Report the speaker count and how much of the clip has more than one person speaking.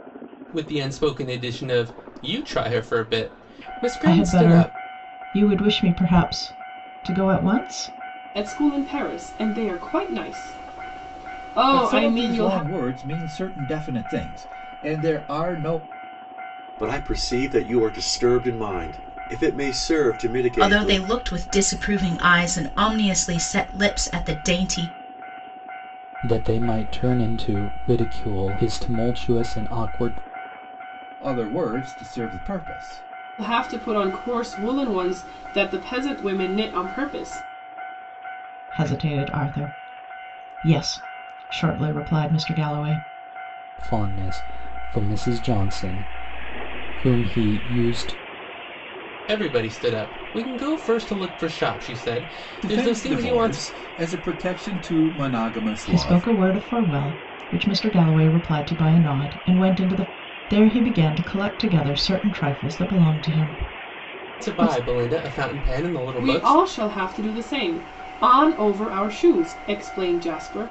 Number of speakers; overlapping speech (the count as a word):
seven, about 7%